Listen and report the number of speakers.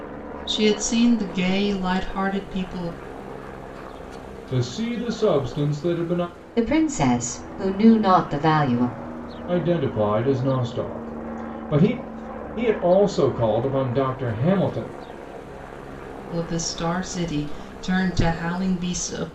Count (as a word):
three